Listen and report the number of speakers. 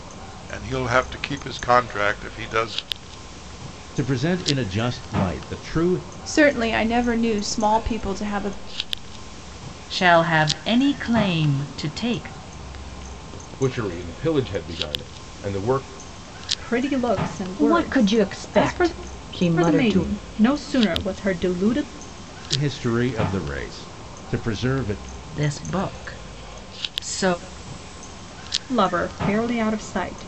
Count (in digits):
7